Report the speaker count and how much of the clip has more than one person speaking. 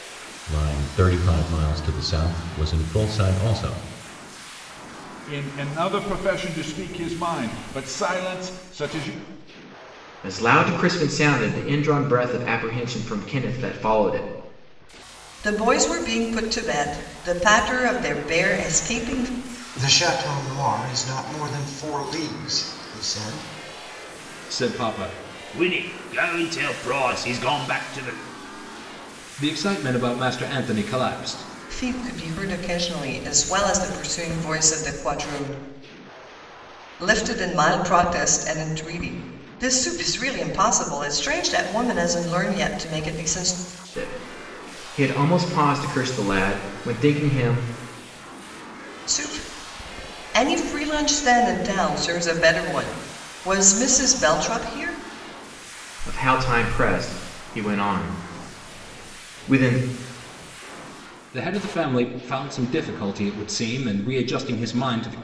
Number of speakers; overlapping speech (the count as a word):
six, no overlap